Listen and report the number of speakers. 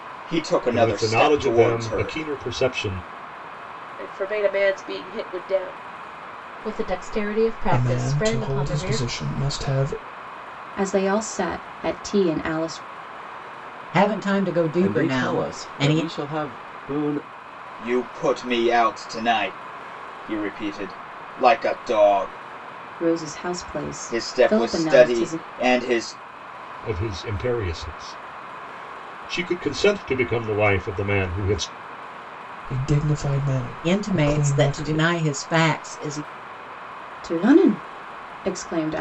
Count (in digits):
8